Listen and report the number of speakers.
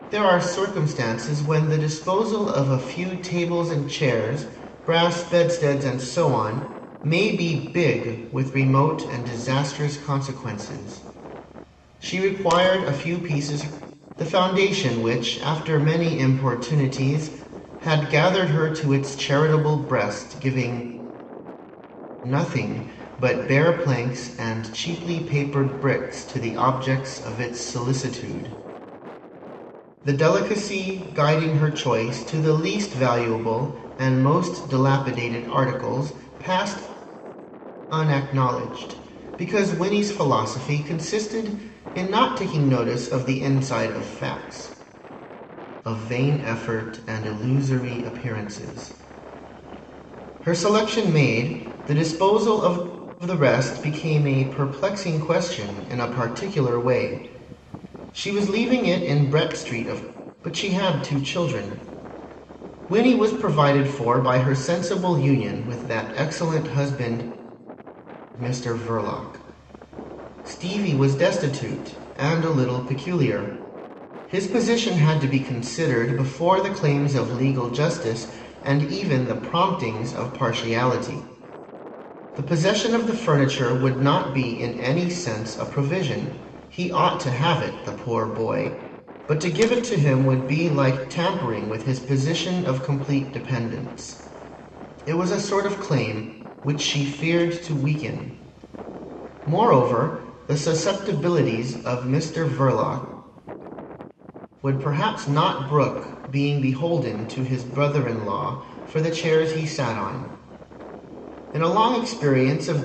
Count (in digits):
1